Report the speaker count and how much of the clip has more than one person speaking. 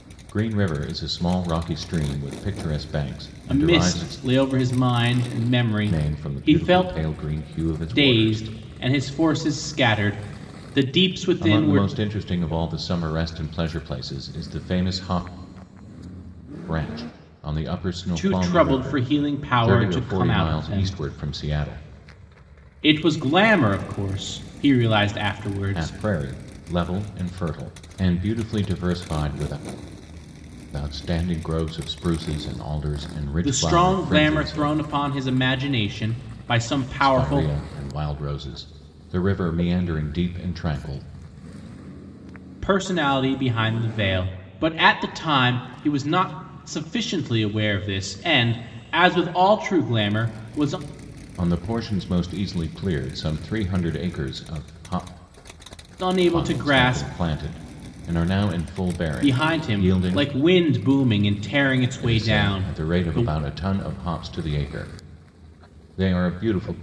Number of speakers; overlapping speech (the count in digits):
2, about 17%